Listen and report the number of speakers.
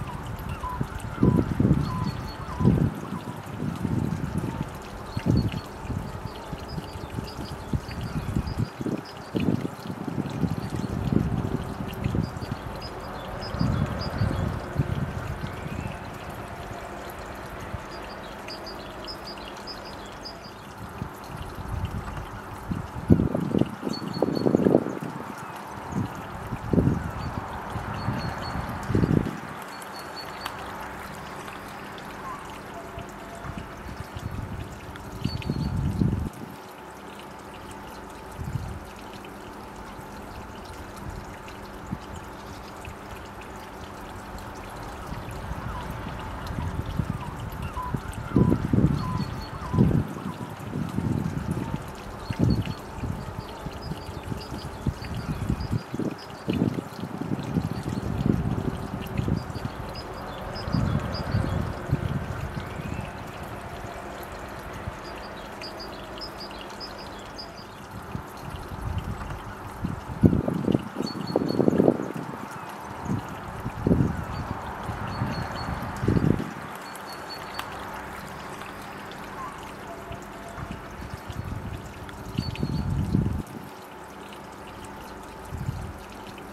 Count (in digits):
0